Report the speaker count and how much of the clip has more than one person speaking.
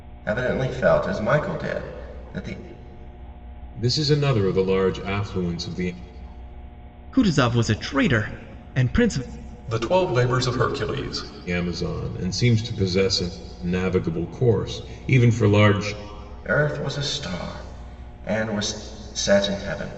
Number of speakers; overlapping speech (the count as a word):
four, no overlap